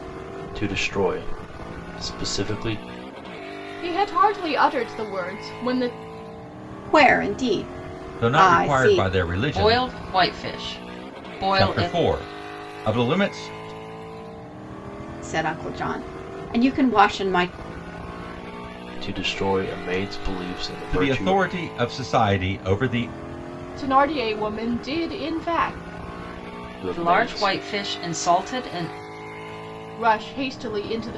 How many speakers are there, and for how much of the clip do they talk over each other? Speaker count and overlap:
5, about 9%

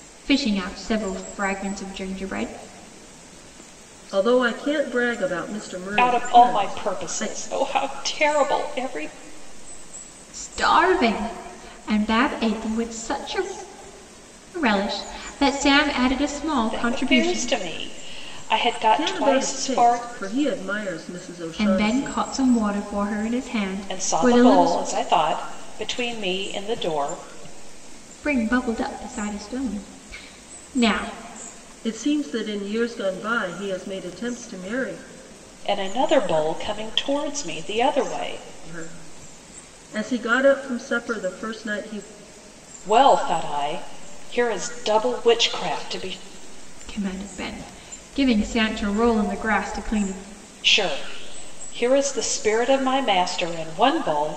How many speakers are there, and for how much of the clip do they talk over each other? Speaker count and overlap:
3, about 9%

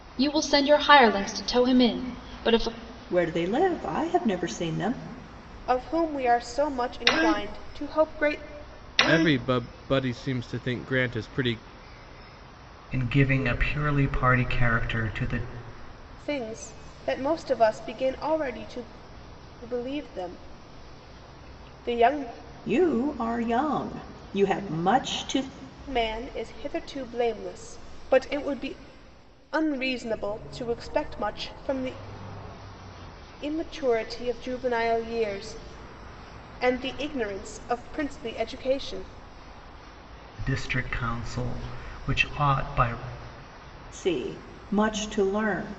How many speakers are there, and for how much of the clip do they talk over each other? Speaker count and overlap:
5, no overlap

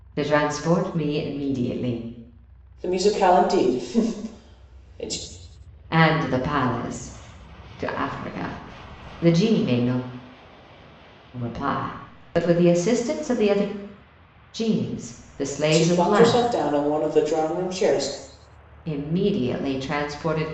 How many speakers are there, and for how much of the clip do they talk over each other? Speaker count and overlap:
2, about 4%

